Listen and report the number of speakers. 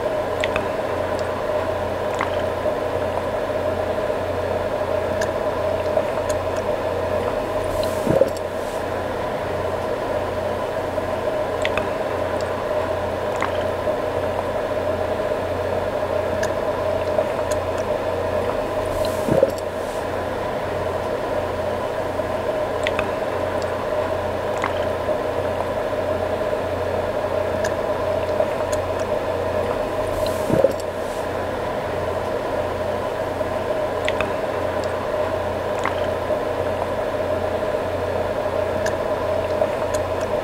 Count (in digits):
0